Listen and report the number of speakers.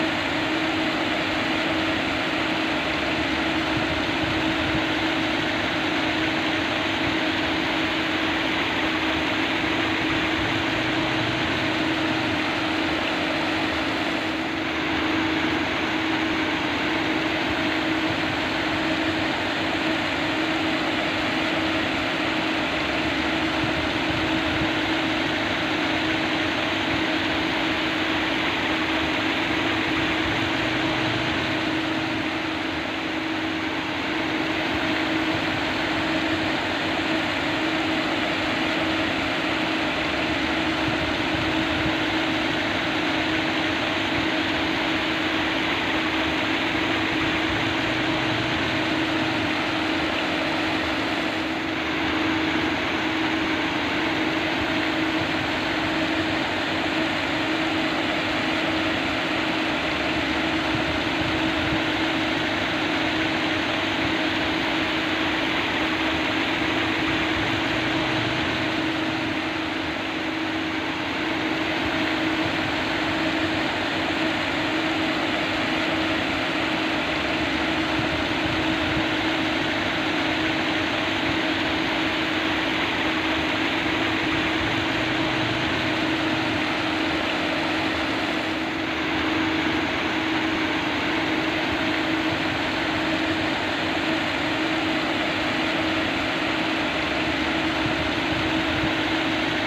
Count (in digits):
0